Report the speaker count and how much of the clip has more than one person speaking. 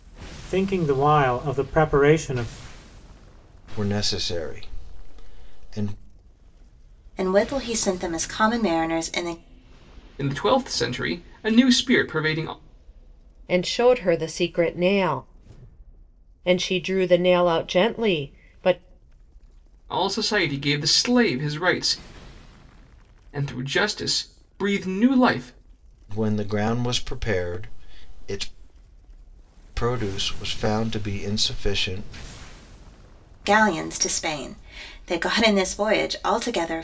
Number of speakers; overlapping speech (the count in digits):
5, no overlap